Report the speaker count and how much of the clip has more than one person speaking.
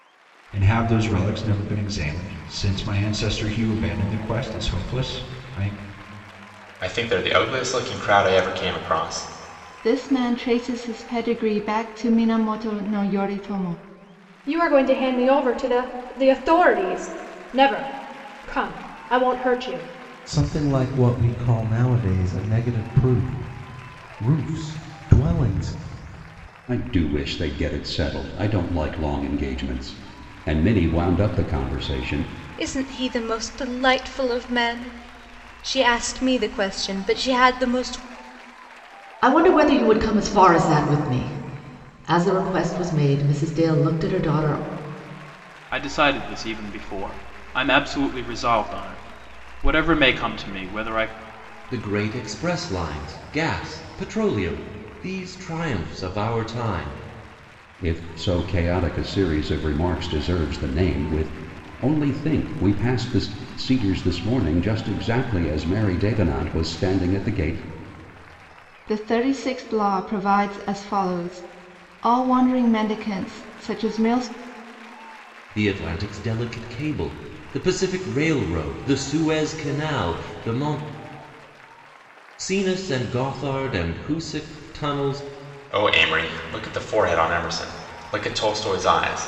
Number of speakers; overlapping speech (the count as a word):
ten, no overlap